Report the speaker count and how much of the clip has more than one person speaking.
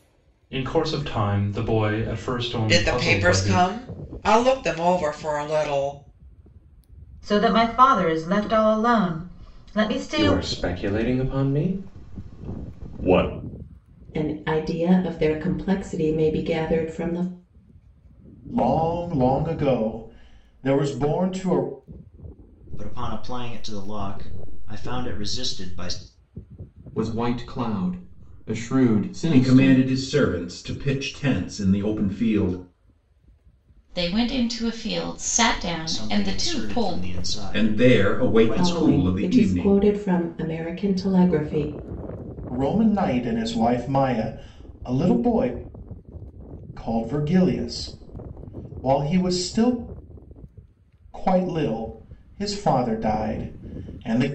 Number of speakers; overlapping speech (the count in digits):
10, about 10%